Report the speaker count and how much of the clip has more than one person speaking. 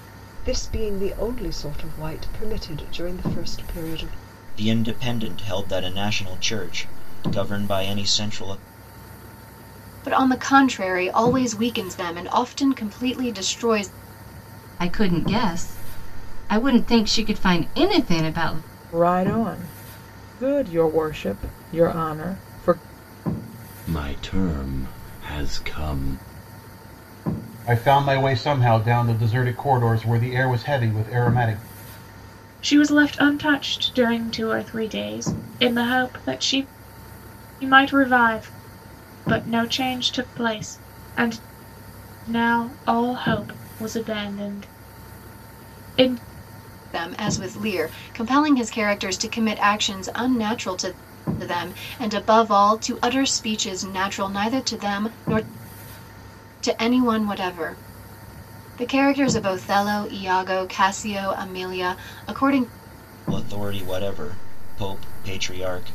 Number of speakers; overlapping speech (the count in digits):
8, no overlap